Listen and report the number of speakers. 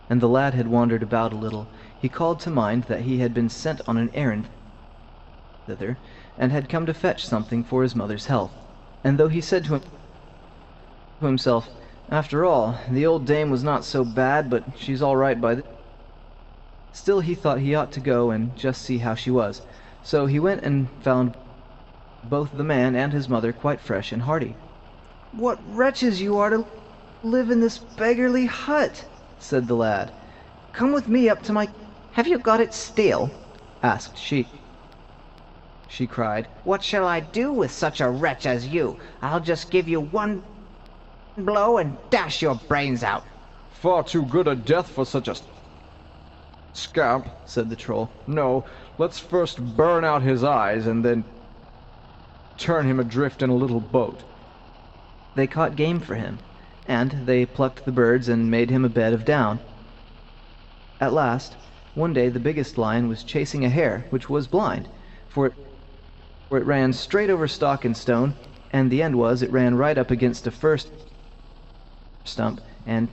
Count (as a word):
one